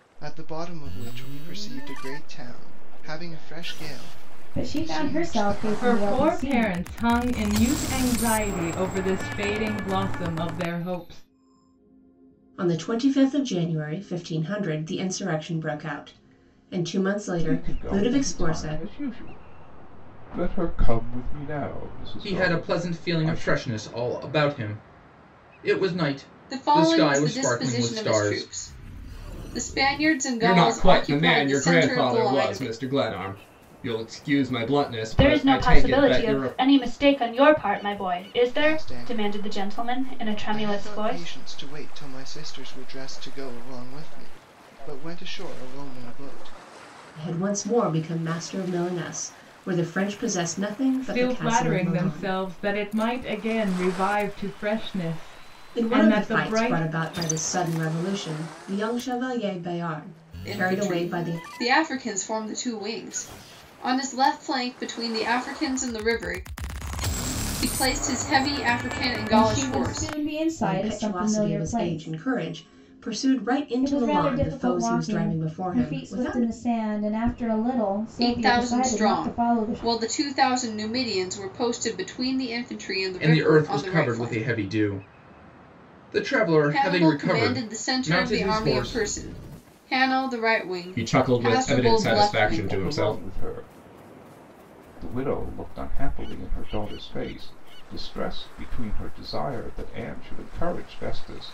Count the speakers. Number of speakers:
9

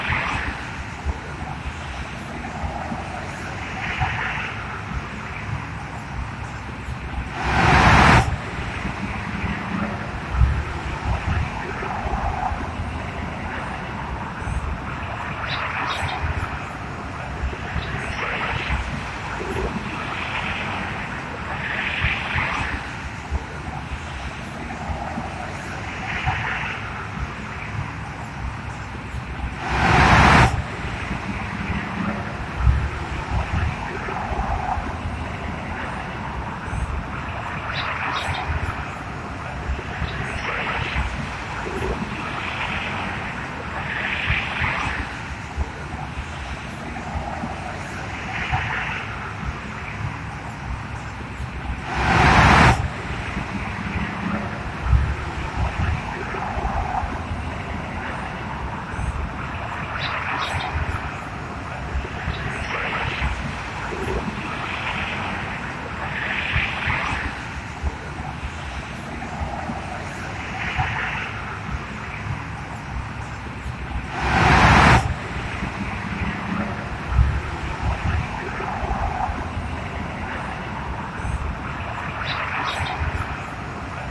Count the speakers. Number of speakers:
0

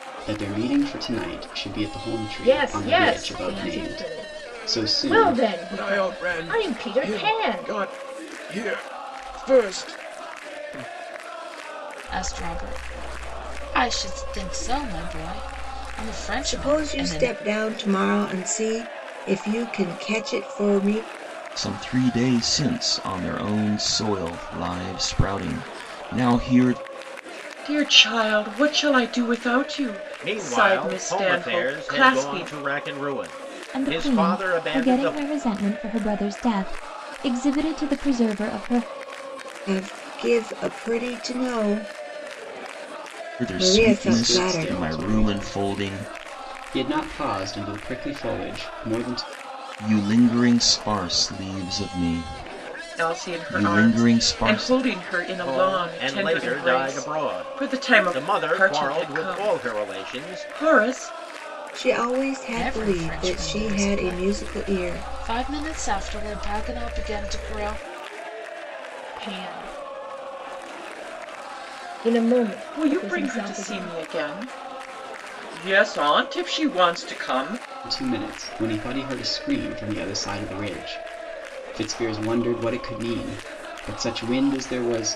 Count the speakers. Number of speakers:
9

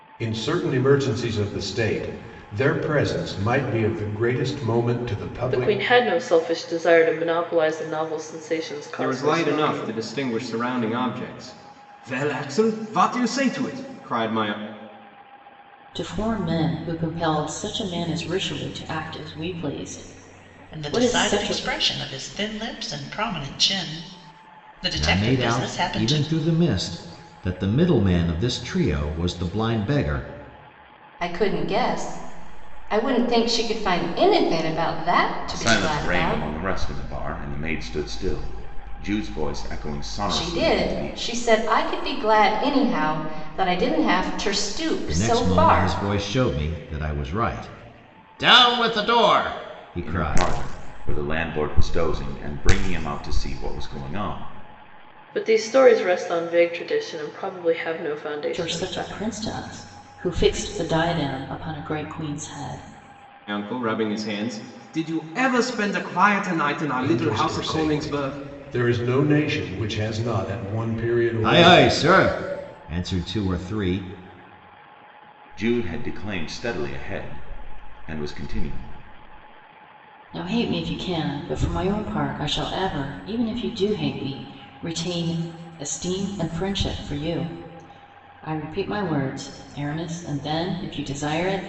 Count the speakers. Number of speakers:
8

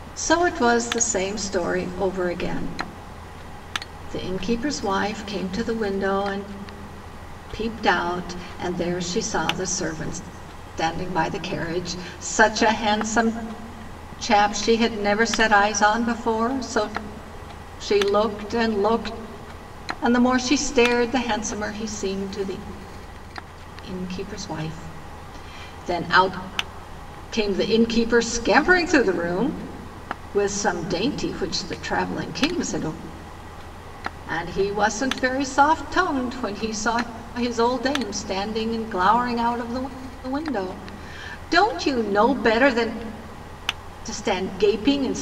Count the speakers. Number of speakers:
1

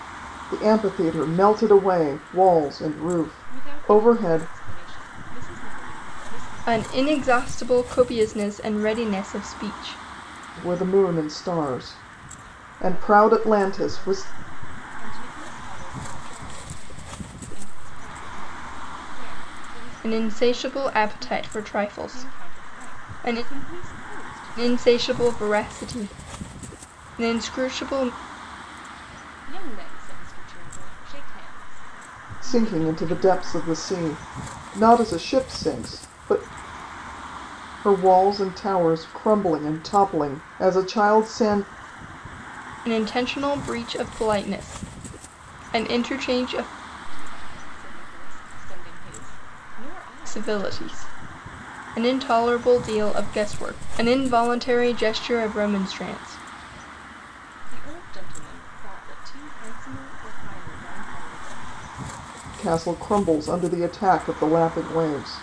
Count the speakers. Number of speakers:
3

